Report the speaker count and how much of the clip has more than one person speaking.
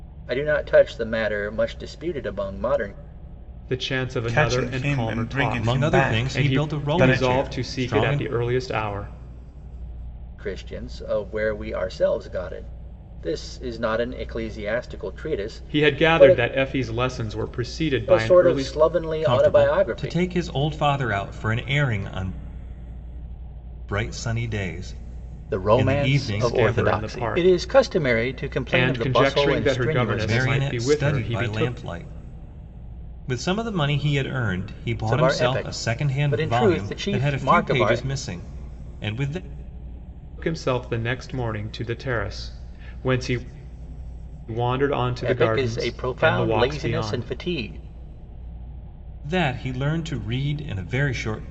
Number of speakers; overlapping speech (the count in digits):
4, about 33%